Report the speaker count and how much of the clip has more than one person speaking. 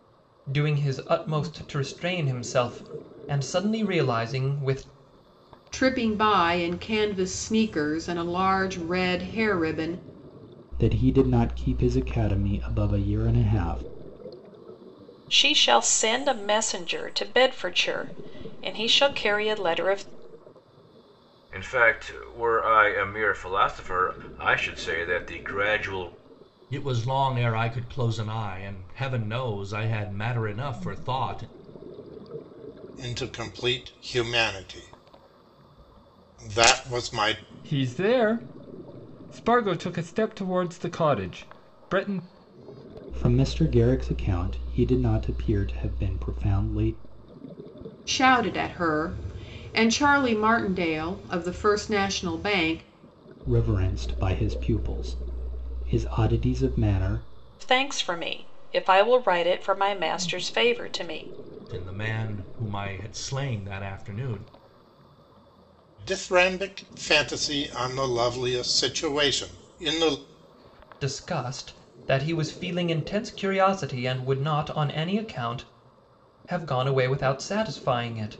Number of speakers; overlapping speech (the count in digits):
8, no overlap